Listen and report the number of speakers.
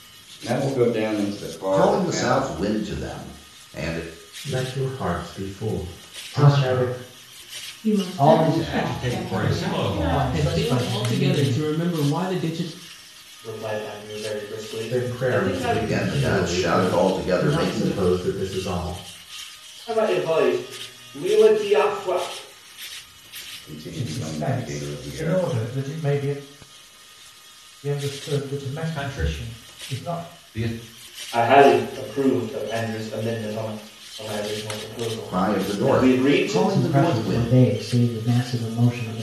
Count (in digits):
9